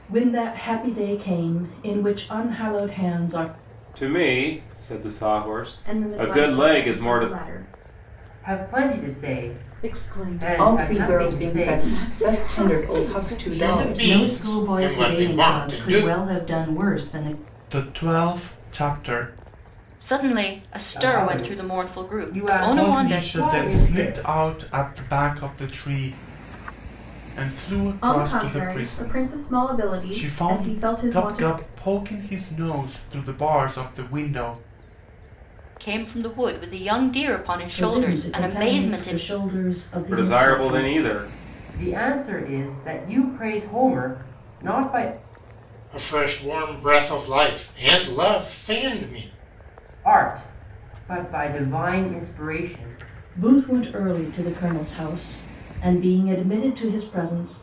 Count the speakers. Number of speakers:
10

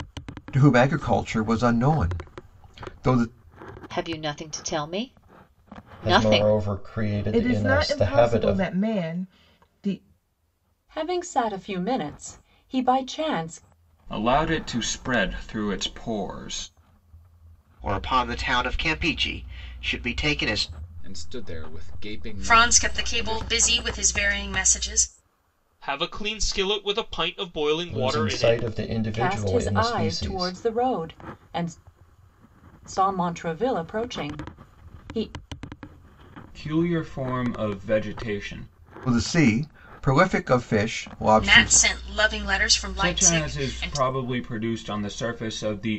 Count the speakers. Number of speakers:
10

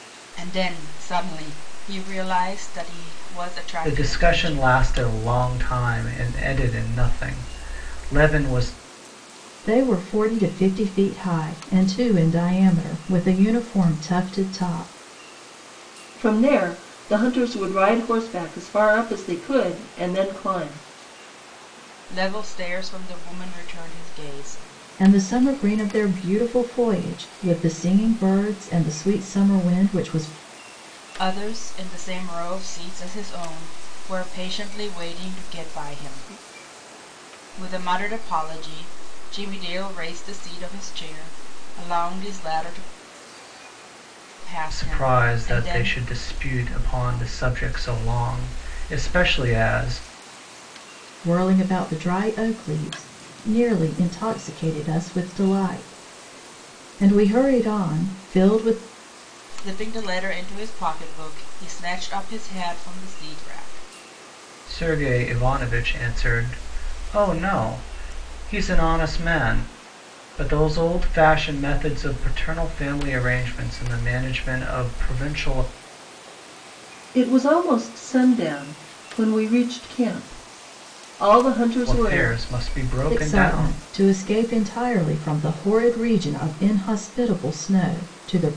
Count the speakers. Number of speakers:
4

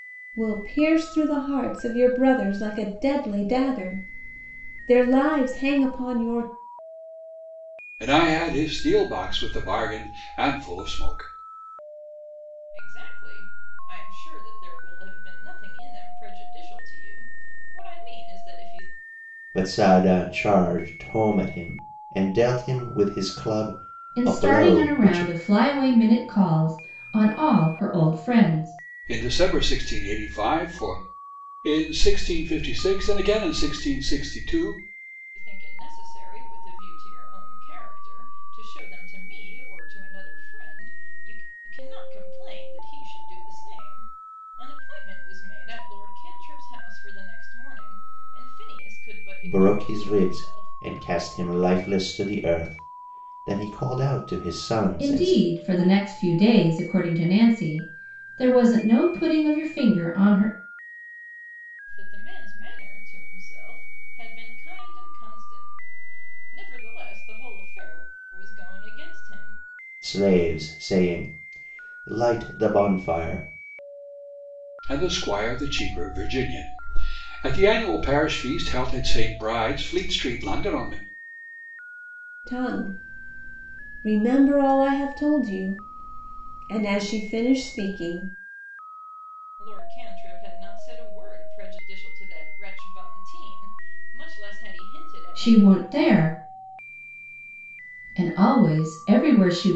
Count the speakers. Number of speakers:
5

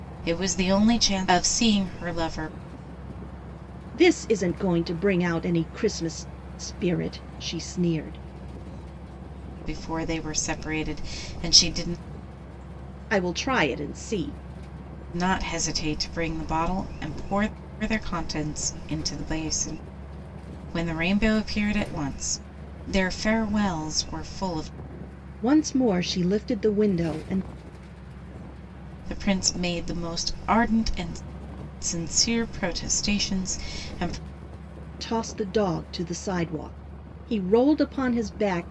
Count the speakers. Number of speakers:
2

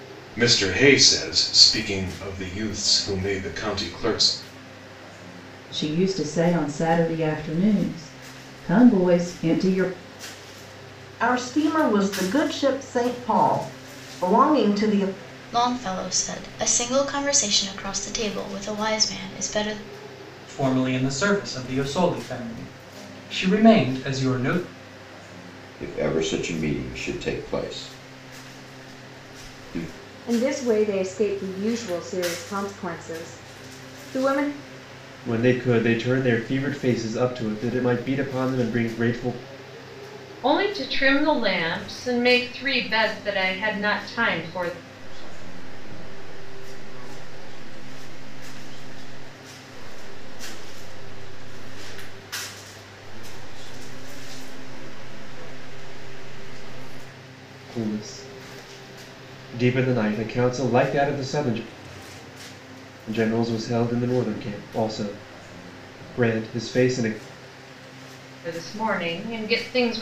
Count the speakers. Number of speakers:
10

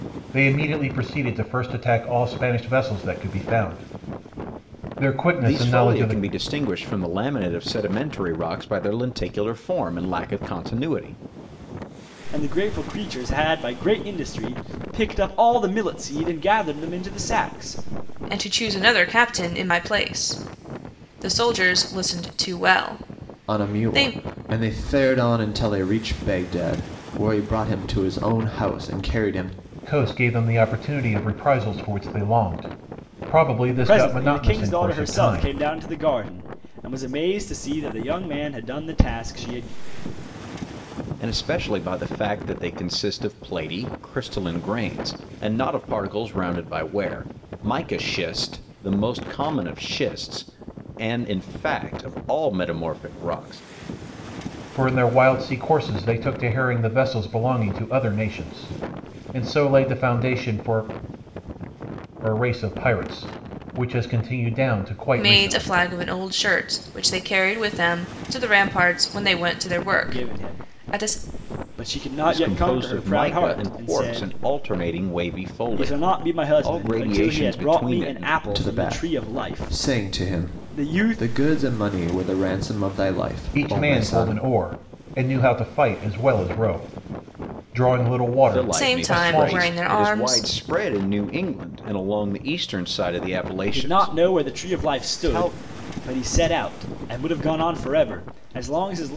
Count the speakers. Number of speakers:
5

